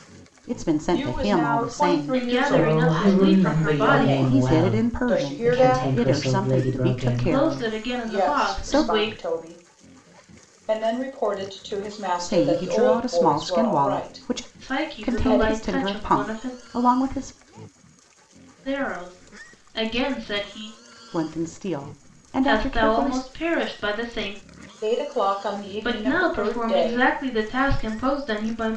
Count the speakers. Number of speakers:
4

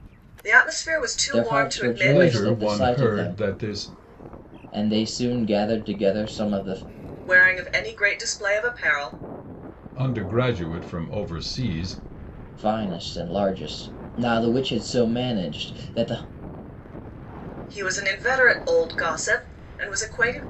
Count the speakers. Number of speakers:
3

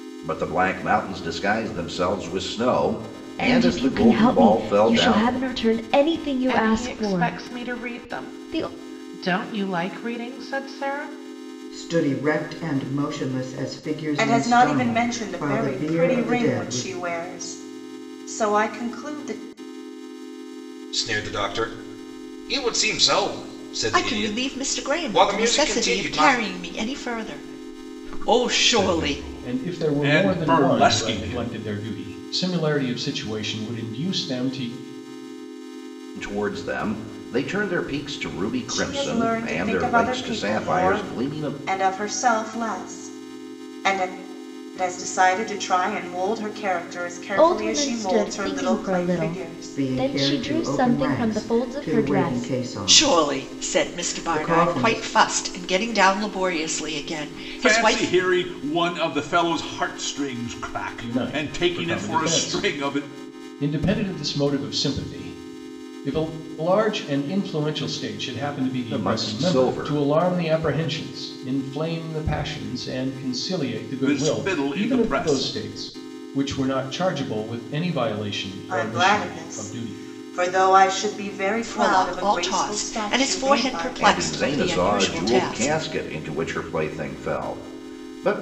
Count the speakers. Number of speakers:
9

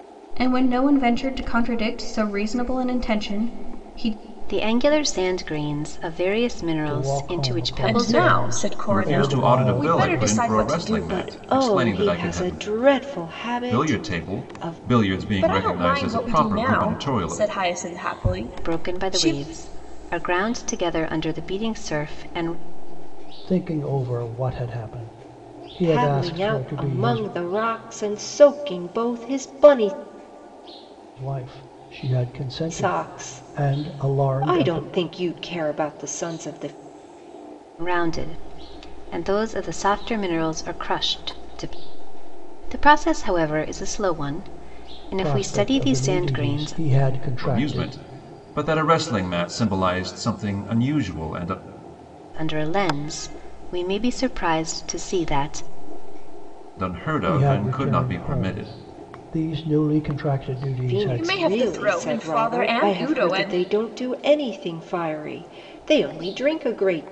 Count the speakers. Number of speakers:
6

